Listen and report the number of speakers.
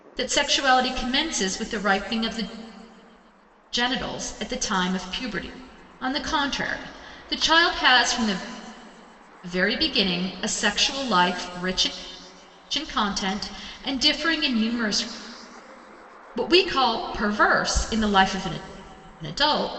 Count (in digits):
1